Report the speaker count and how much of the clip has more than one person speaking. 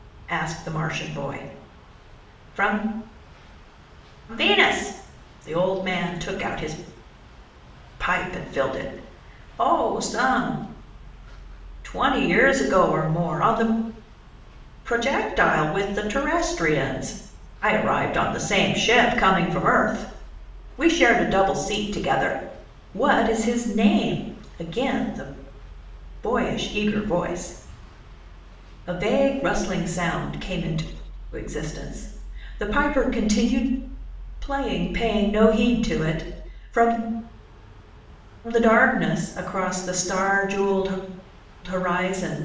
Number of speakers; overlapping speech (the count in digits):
1, no overlap